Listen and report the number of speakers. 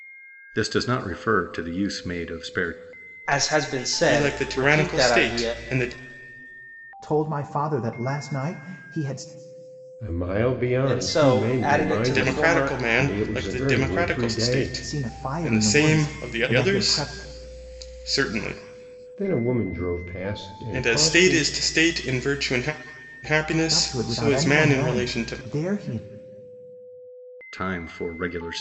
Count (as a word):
five